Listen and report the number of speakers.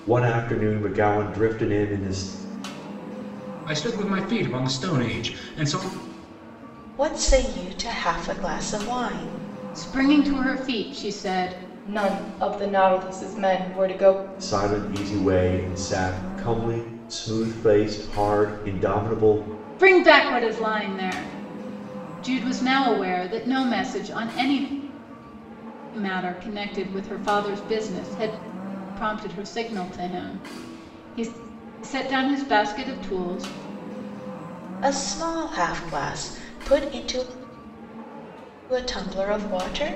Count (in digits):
5